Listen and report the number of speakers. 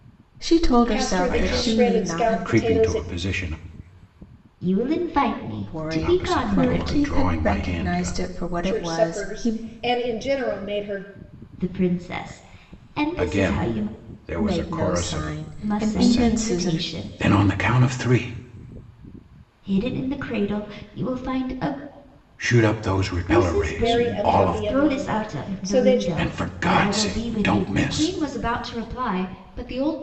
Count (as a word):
four